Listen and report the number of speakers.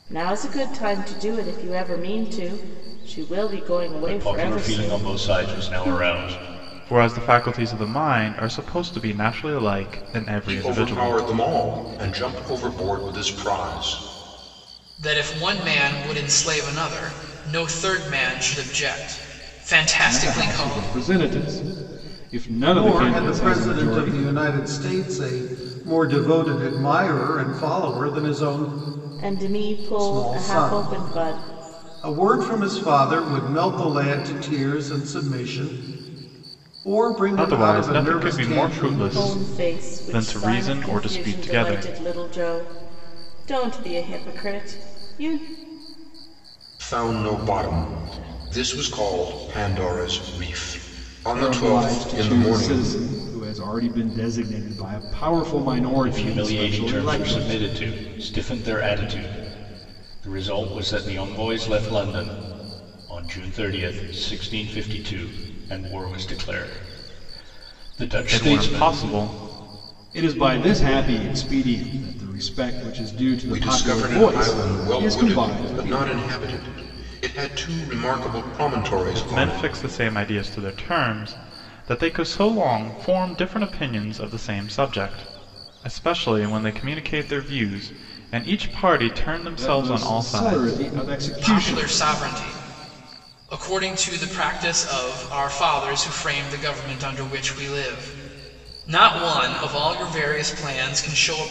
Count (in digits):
7